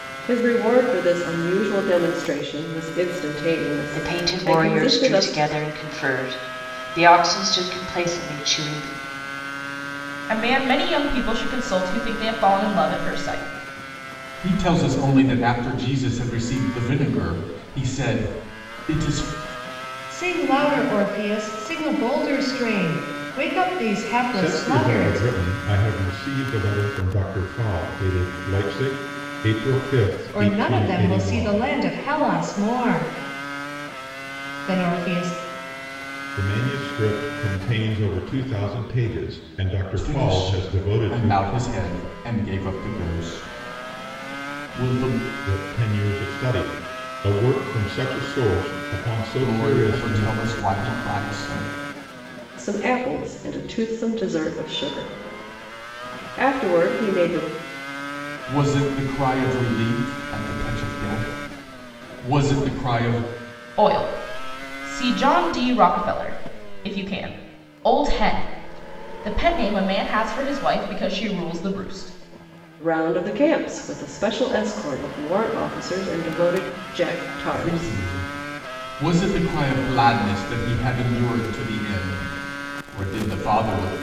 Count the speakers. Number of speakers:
six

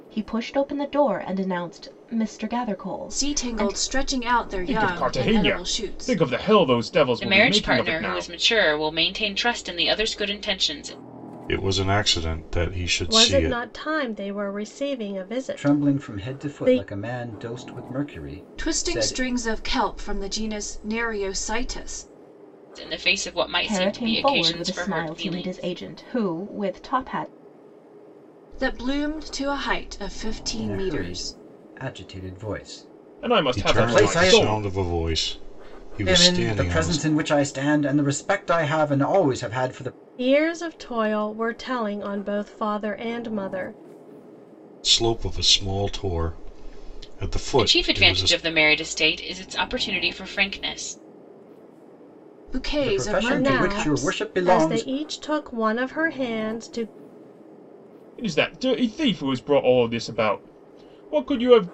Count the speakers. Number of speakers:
seven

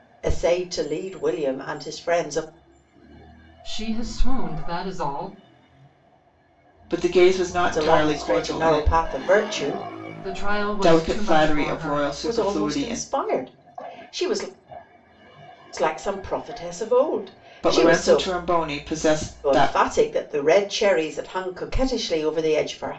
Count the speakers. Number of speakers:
three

